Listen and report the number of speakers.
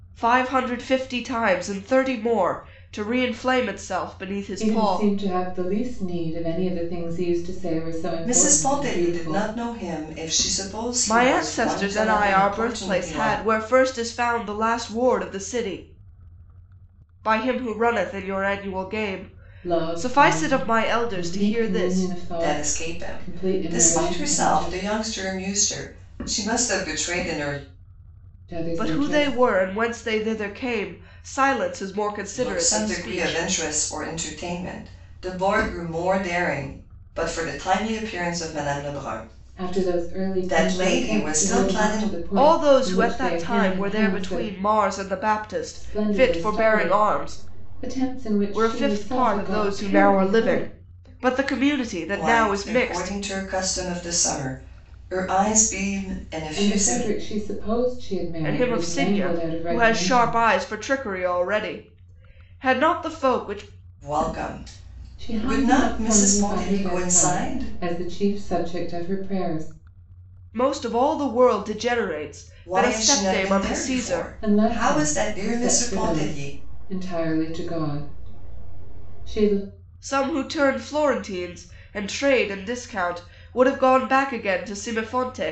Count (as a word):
three